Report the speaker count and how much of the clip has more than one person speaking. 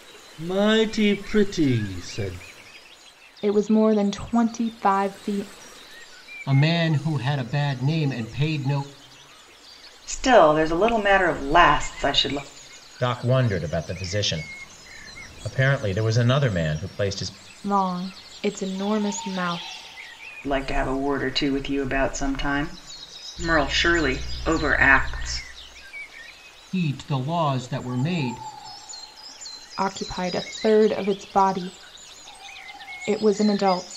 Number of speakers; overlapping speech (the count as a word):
five, no overlap